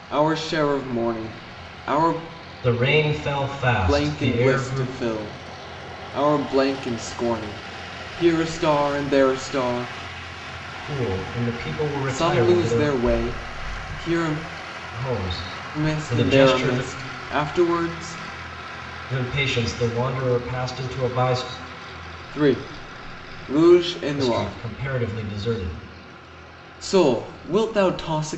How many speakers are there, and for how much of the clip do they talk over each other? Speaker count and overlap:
2, about 12%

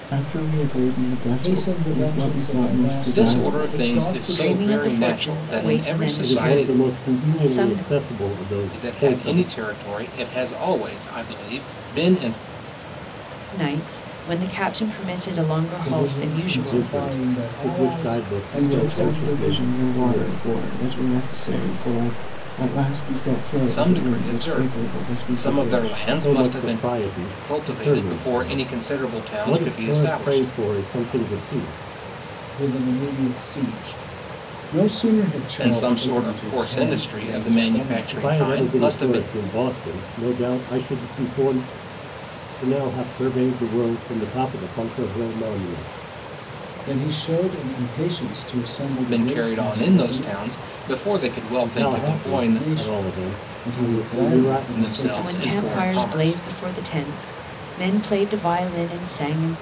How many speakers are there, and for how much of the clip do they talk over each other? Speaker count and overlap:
5, about 47%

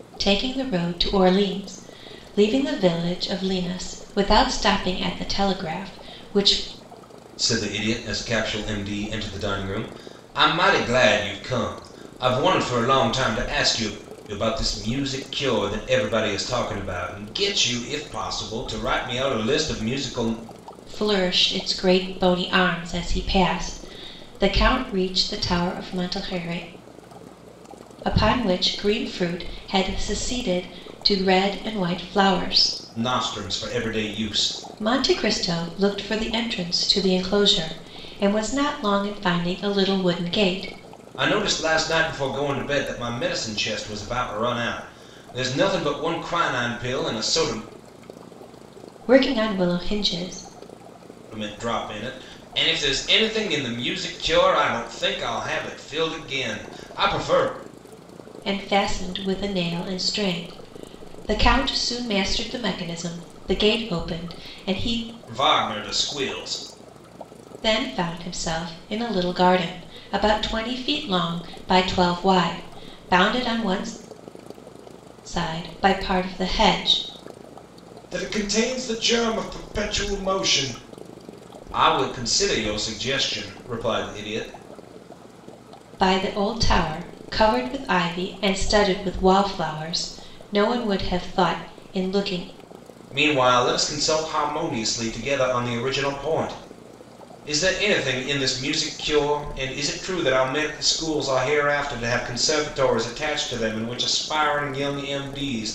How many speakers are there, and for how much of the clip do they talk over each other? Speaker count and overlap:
2, no overlap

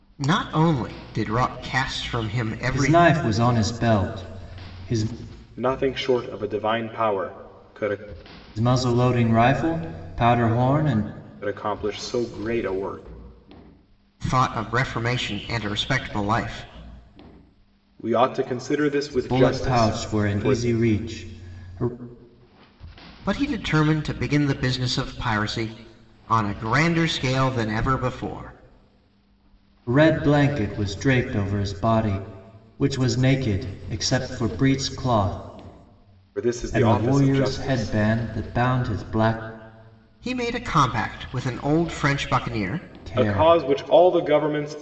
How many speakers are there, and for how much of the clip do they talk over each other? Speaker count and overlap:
3, about 8%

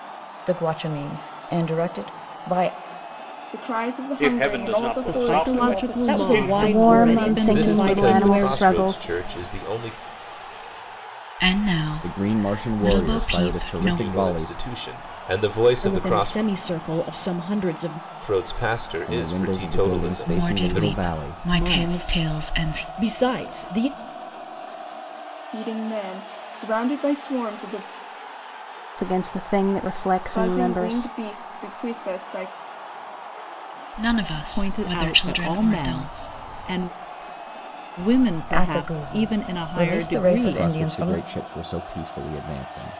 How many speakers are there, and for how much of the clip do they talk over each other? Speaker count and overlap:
9, about 40%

